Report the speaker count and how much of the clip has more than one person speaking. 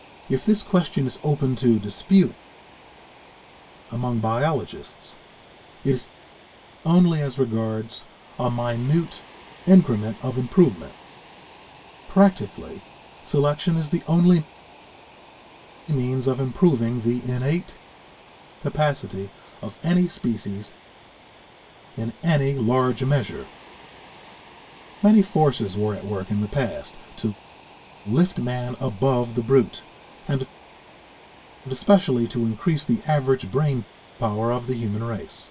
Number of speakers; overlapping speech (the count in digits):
1, no overlap